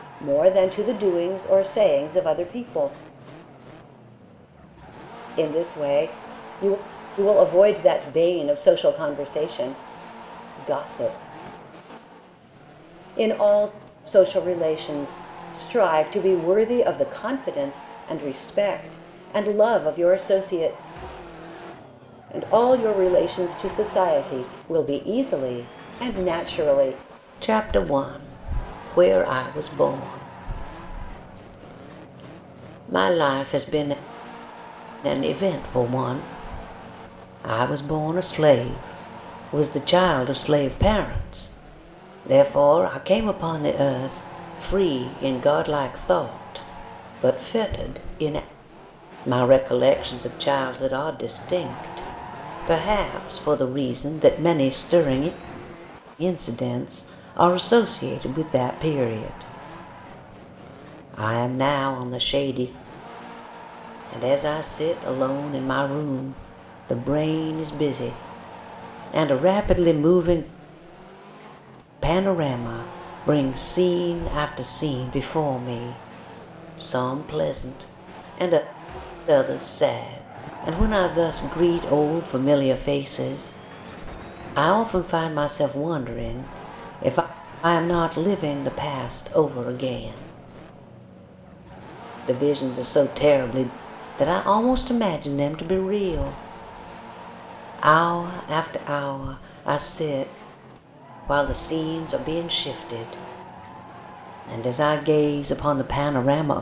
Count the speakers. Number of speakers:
one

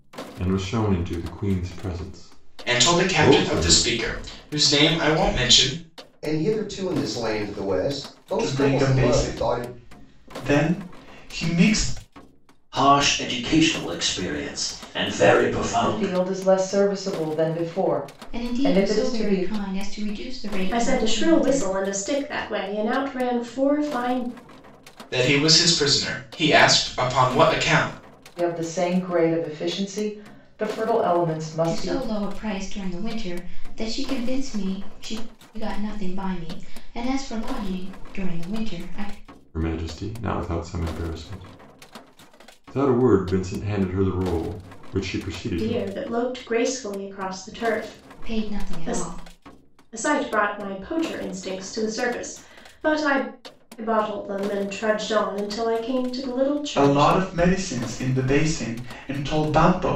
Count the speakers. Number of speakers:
eight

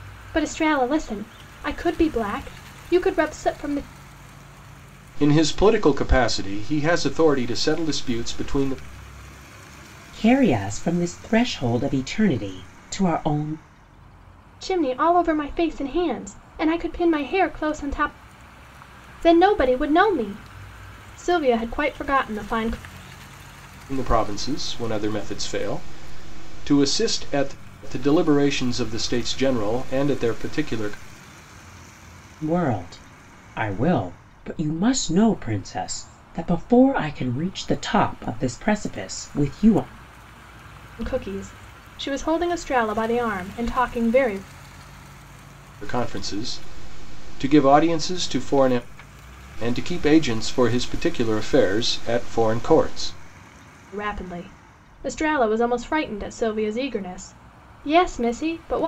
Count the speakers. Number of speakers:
three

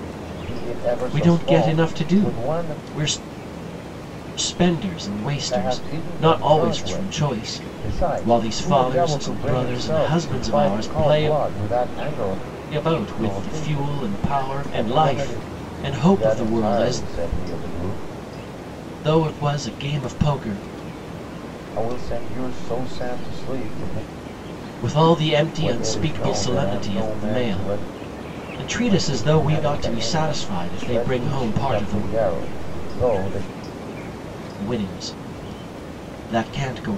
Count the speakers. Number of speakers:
two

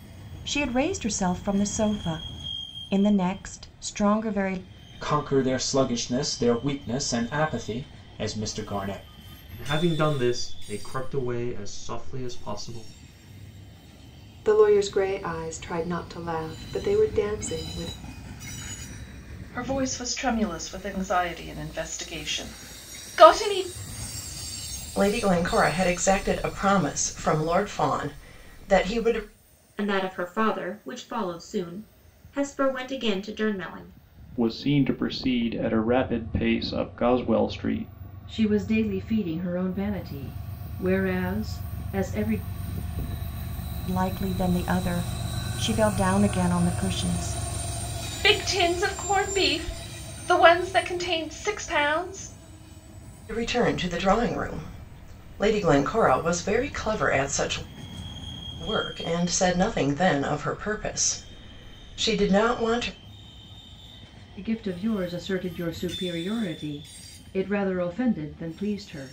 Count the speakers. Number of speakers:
nine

